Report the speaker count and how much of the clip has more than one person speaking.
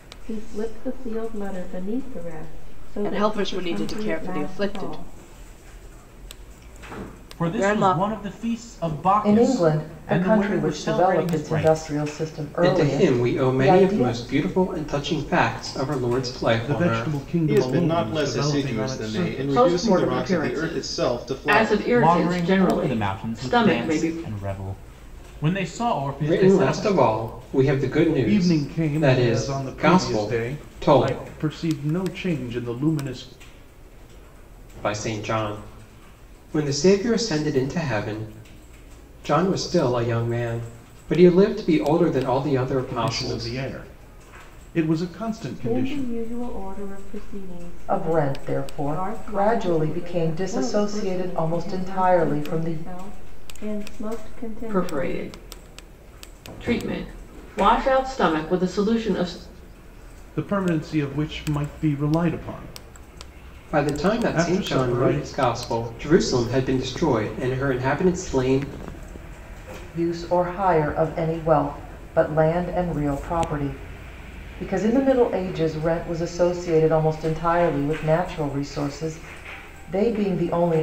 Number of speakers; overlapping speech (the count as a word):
eight, about 33%